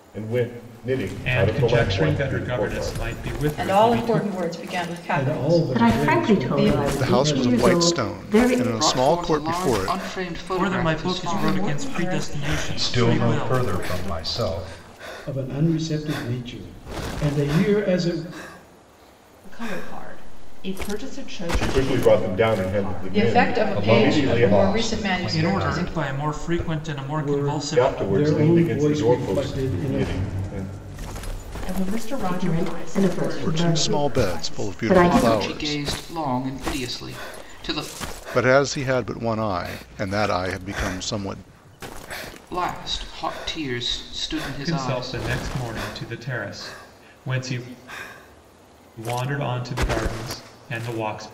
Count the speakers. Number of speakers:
10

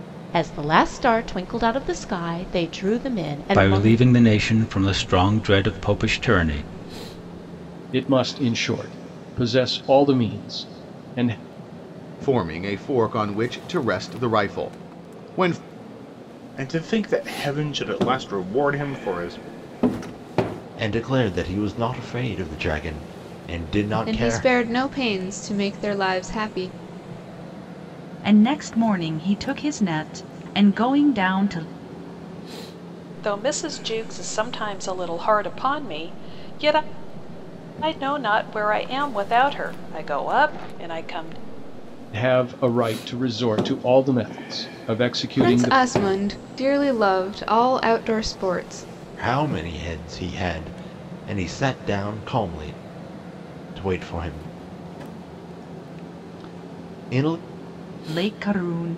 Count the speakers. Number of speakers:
9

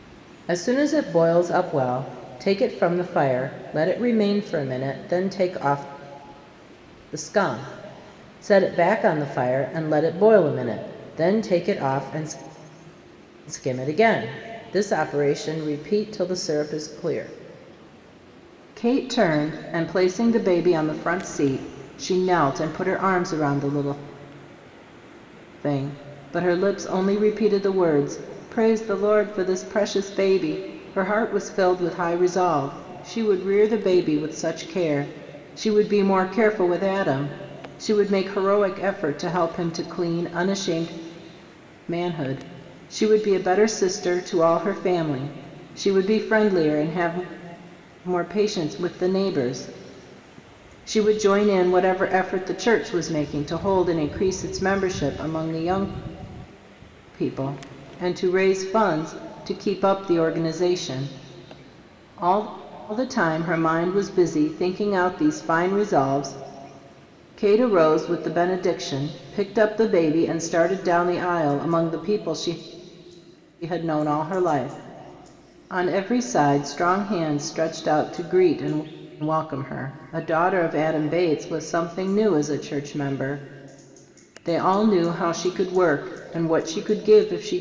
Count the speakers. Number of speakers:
1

